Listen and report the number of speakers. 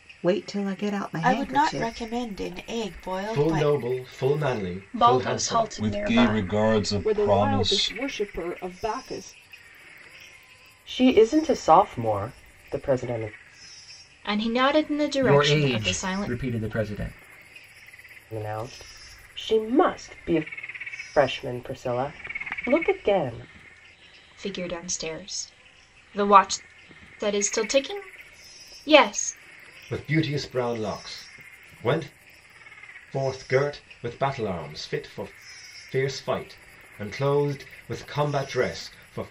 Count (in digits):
9